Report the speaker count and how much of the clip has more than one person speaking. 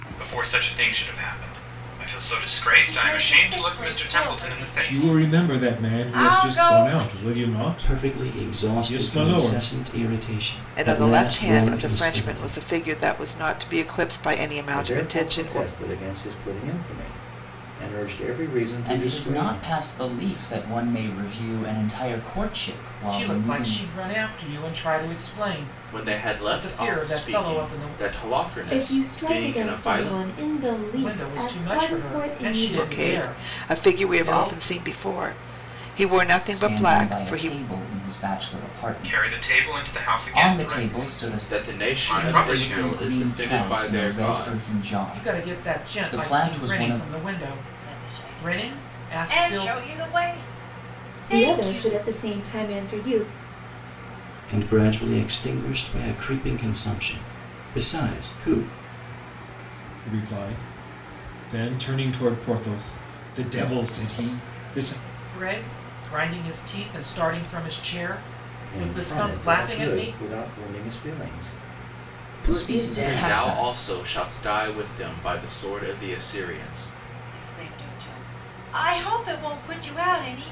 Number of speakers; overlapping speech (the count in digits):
10, about 41%